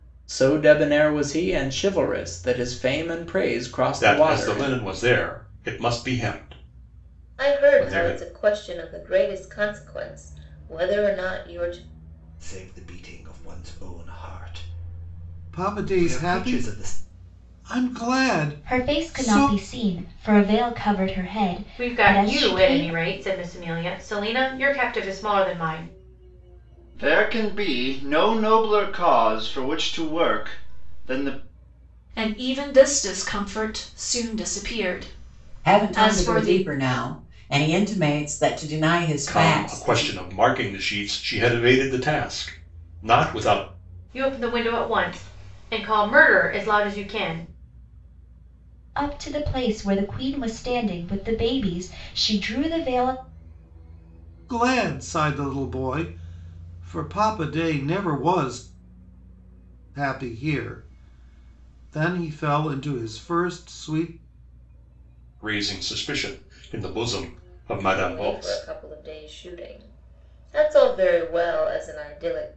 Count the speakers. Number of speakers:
10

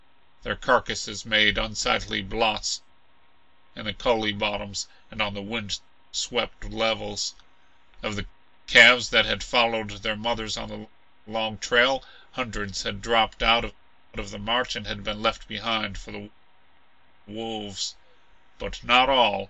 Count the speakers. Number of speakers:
1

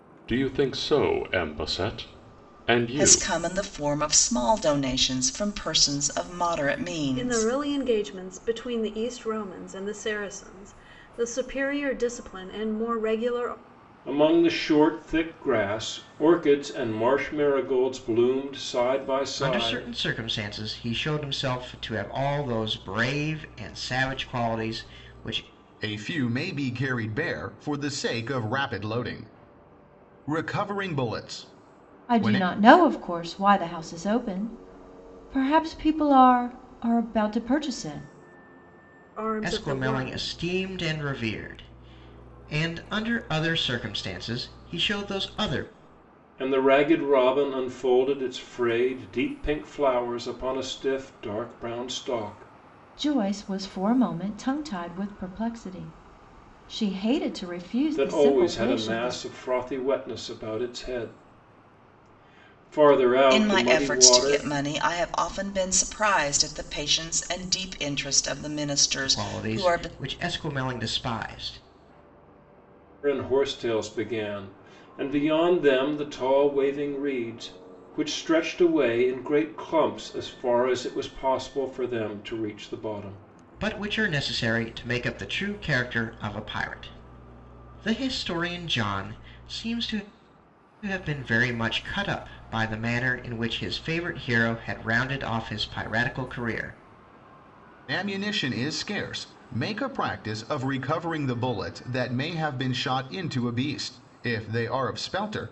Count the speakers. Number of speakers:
7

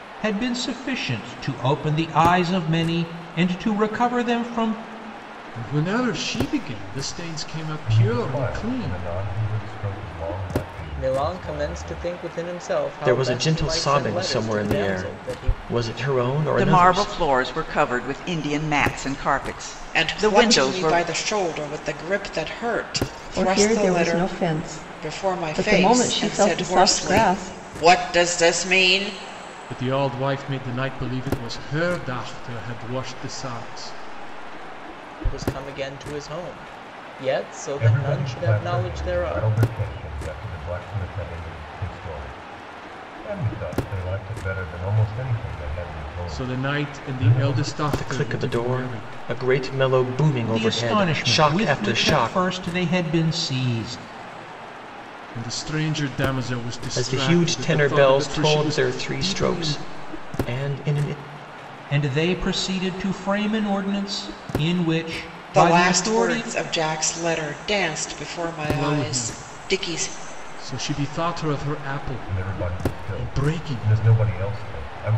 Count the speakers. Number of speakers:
8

